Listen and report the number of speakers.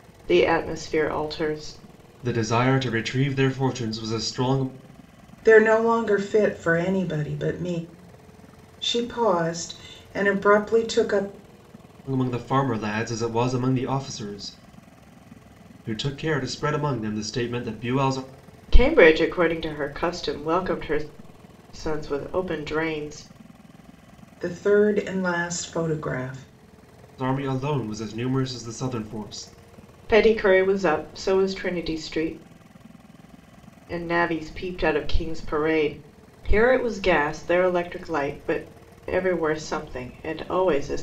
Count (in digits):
3